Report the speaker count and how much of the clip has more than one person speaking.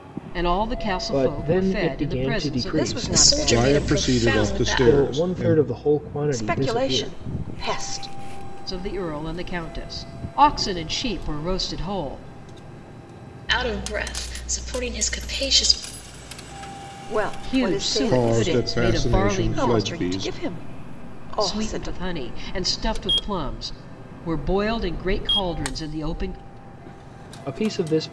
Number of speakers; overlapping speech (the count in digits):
5, about 32%